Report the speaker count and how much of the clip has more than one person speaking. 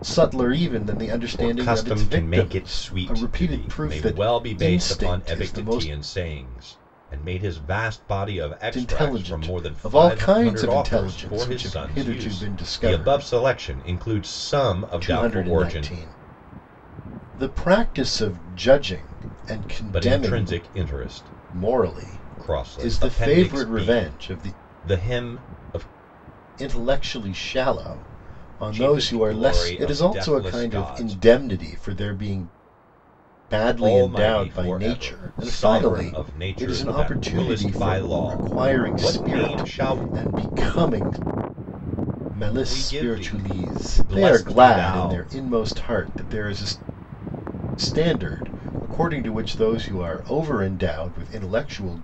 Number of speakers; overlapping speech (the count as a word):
two, about 47%